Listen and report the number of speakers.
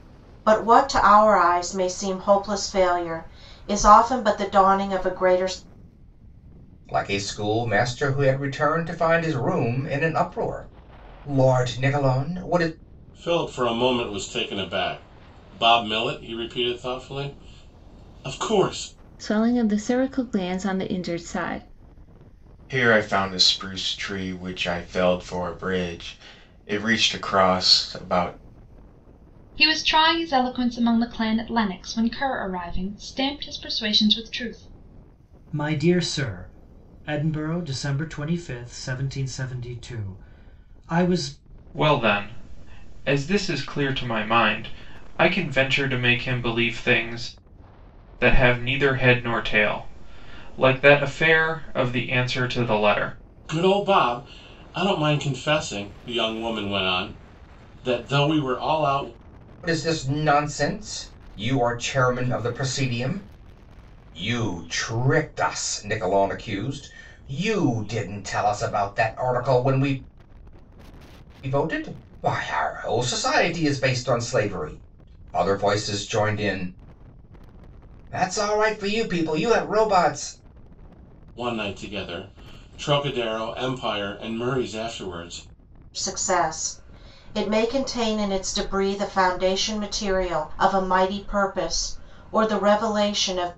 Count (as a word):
eight